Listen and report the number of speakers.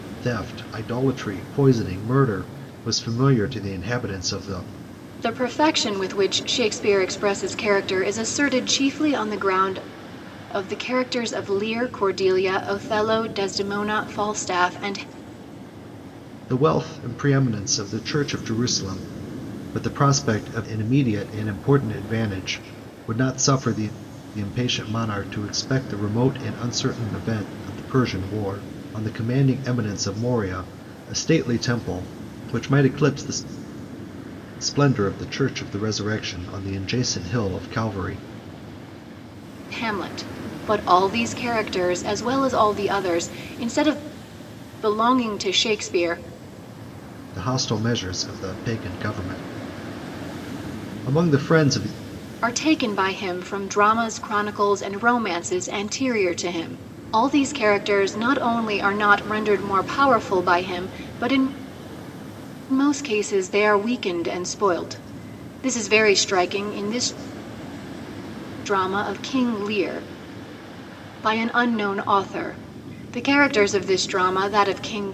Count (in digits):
2